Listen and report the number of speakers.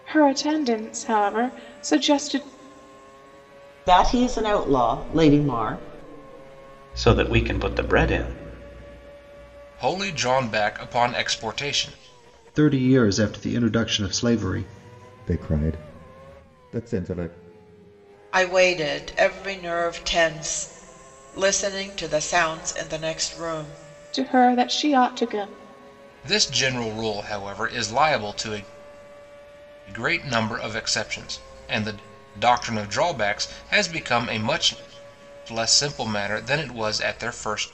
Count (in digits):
7